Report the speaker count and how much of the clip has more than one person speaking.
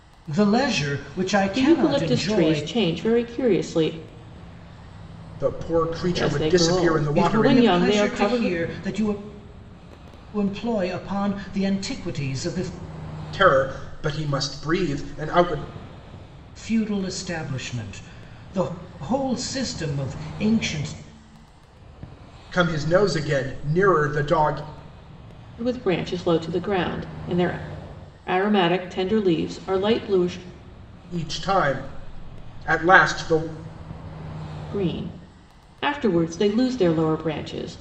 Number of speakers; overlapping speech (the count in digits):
3, about 9%